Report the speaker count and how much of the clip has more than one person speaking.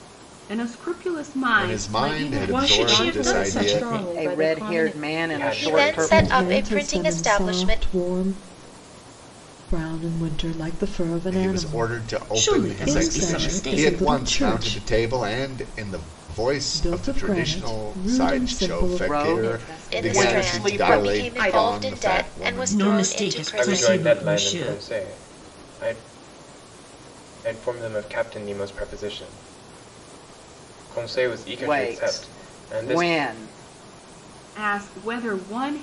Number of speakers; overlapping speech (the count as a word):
eight, about 52%